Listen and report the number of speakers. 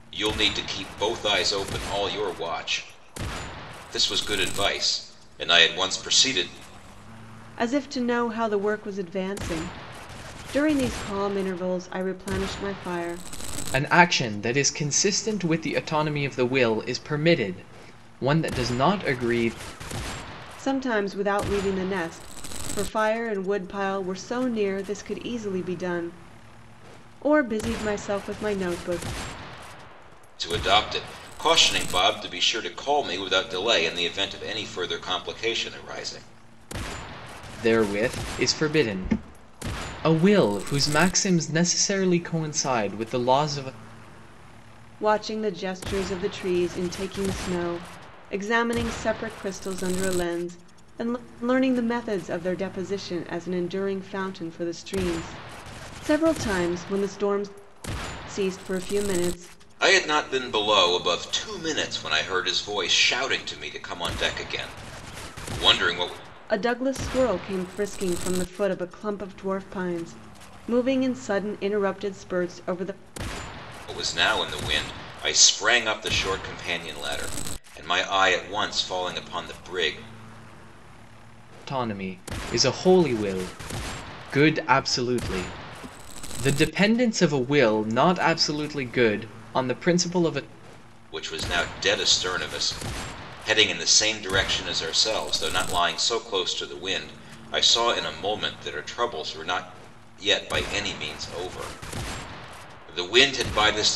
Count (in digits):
3